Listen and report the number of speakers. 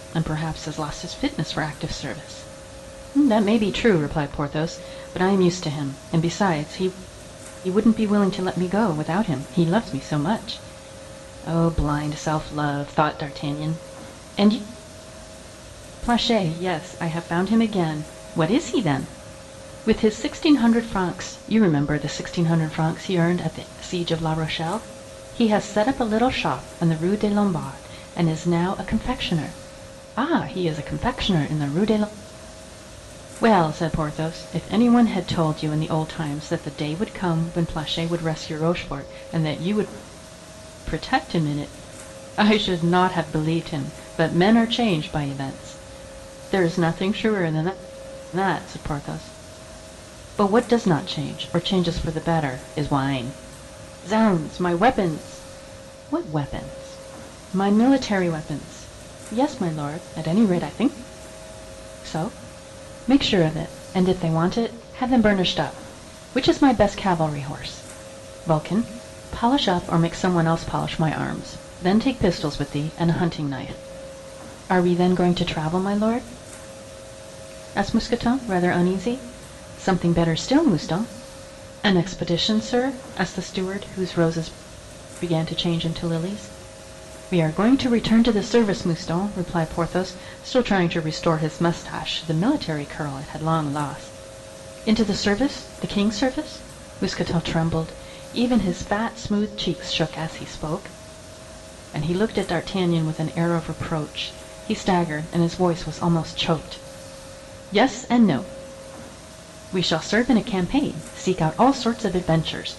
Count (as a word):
one